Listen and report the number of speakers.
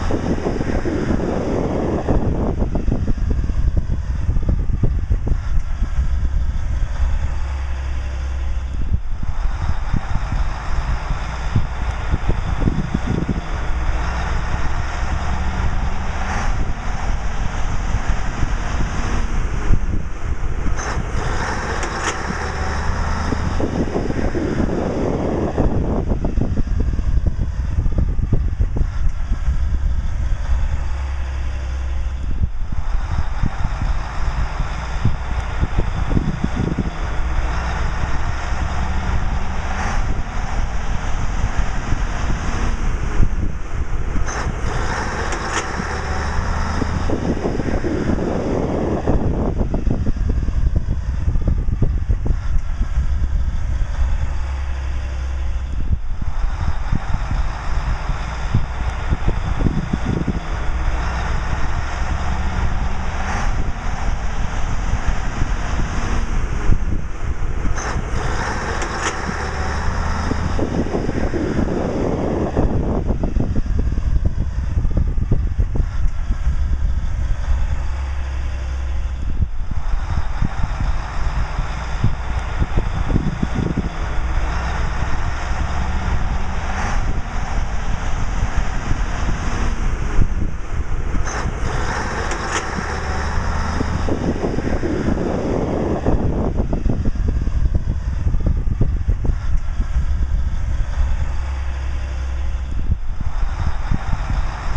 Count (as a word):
zero